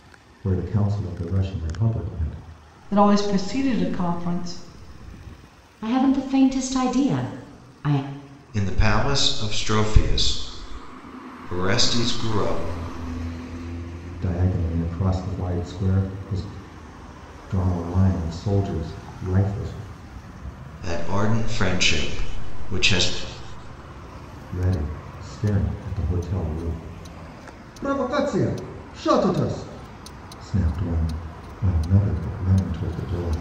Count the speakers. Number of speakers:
4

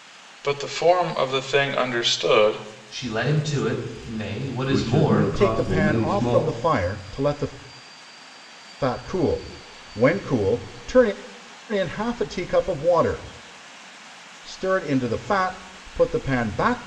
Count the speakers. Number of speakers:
4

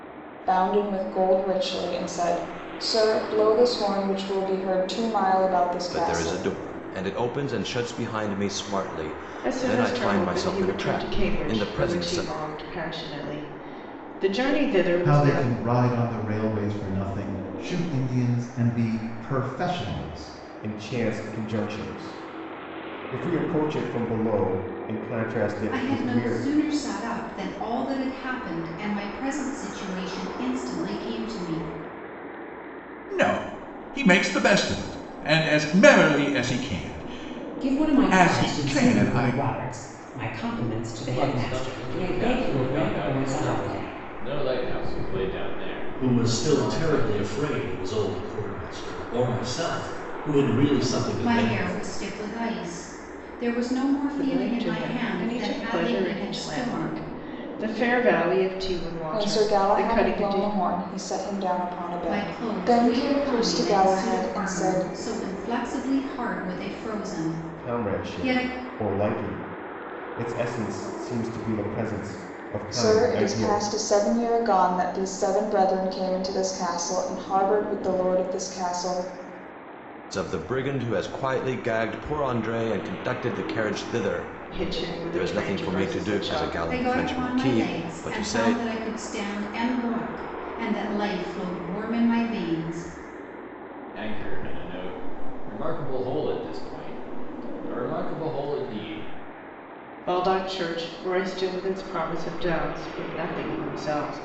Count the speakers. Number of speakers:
10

